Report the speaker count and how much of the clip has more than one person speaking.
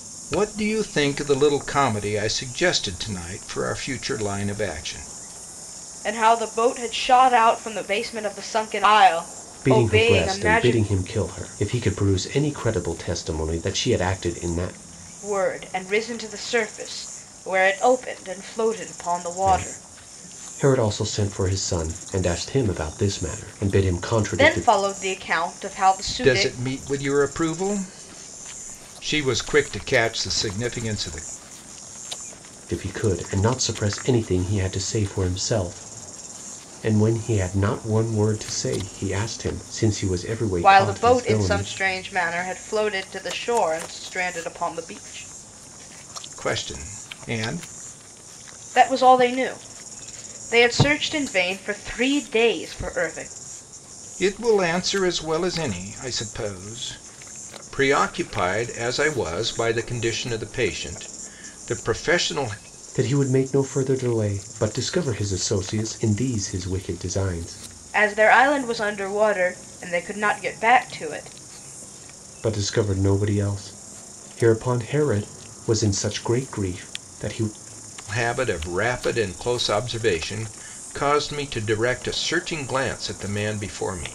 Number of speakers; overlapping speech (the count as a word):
three, about 4%